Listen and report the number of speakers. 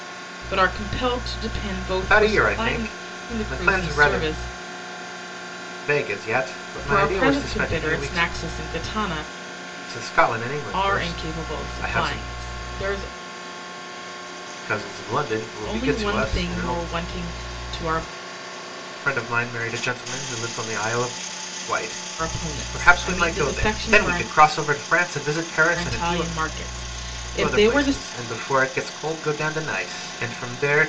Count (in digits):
2